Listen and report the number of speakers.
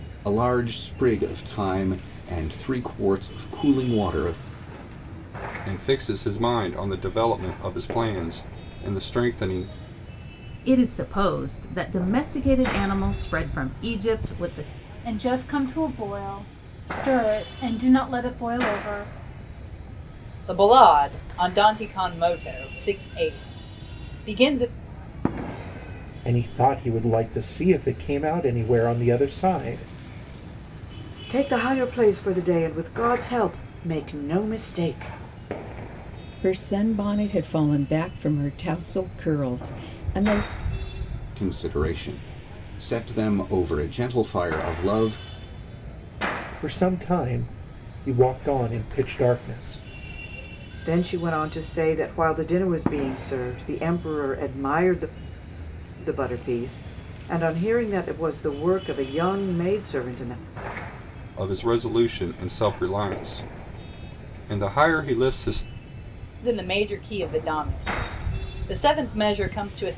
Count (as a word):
eight